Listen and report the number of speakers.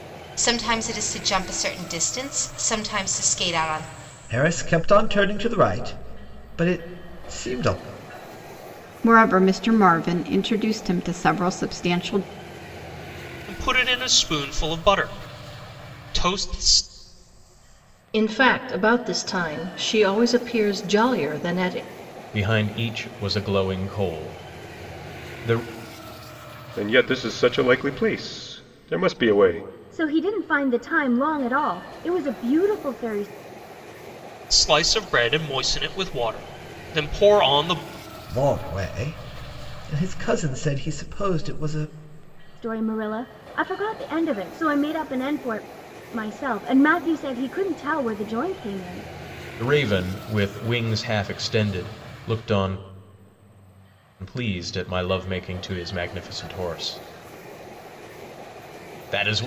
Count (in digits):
8